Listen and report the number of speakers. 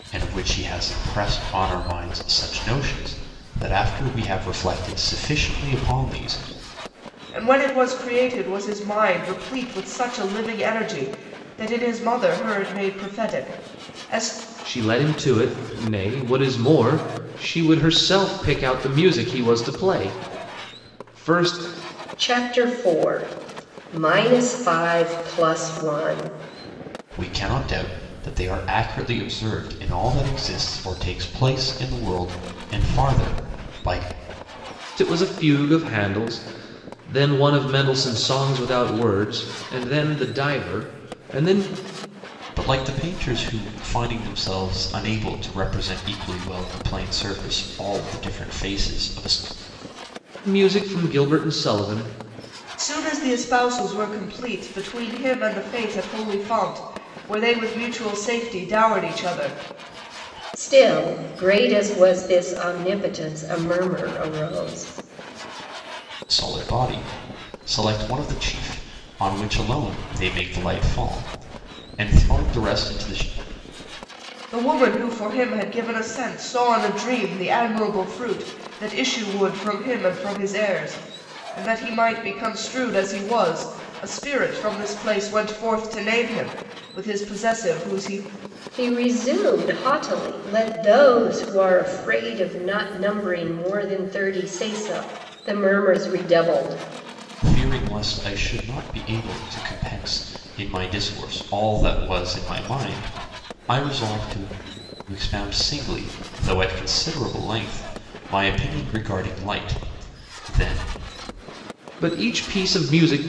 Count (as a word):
four